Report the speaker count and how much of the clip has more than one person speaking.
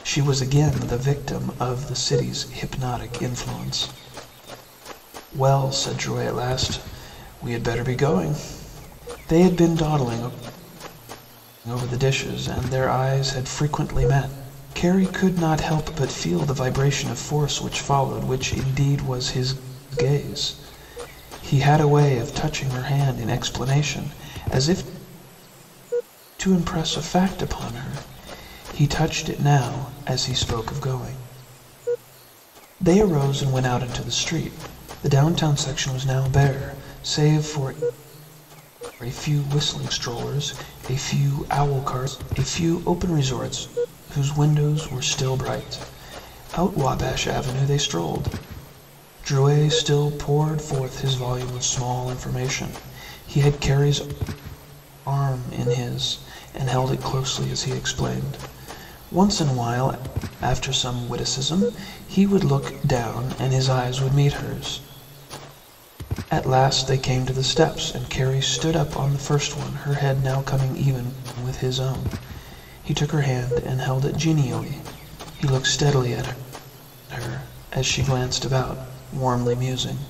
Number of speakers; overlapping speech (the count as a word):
one, no overlap